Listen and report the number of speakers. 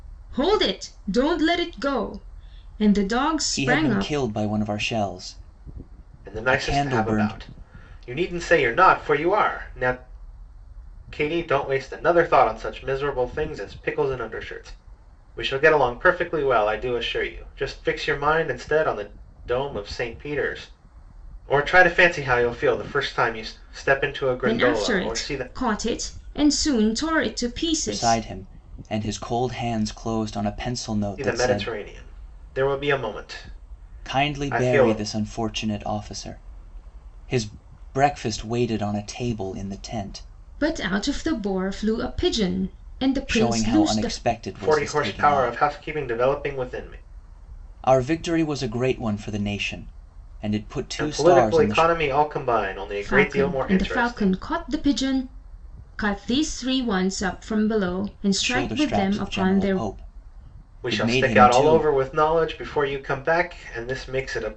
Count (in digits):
3